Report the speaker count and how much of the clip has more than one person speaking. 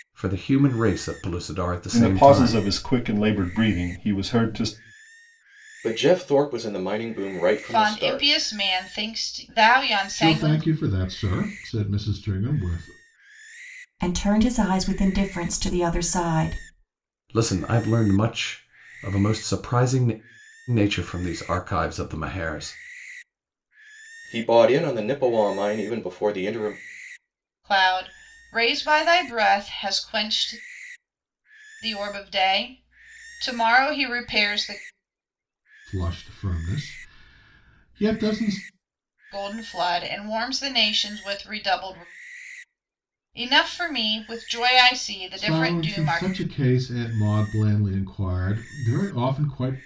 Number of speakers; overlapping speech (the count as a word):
six, about 6%